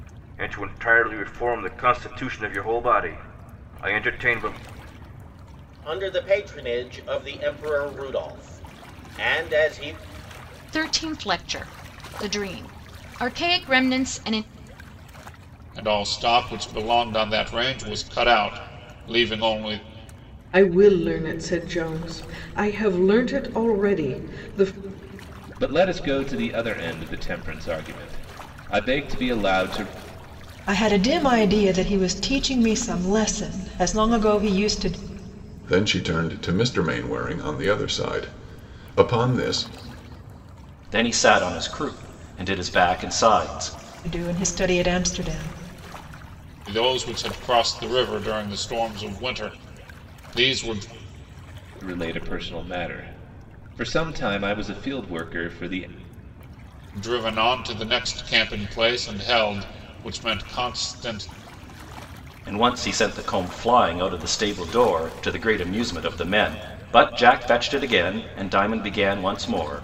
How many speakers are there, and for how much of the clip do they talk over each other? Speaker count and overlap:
nine, no overlap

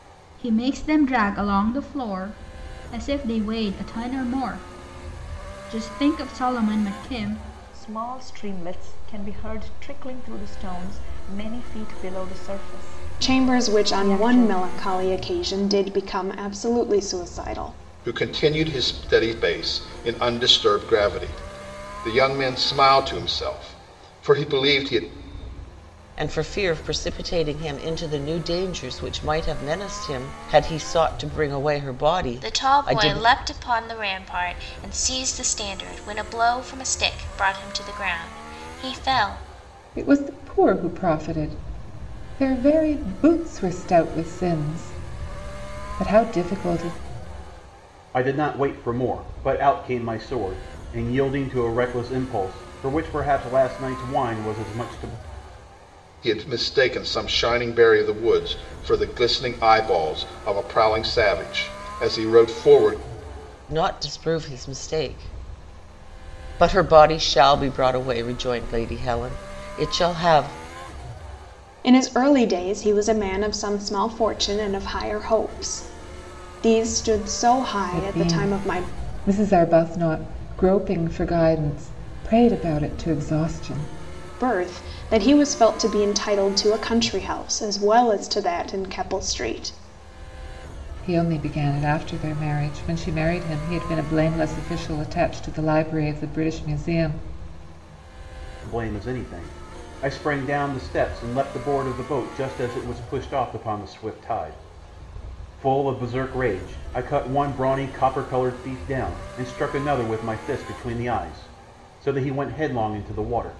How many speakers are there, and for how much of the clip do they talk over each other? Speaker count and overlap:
eight, about 3%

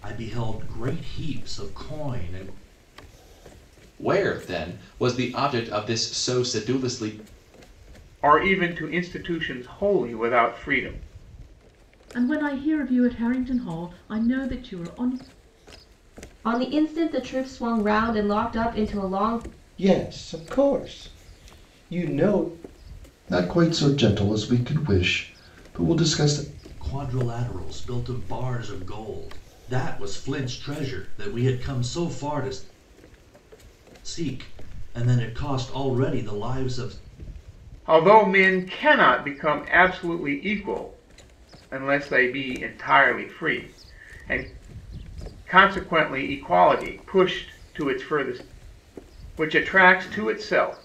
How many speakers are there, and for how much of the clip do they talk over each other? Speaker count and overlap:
seven, no overlap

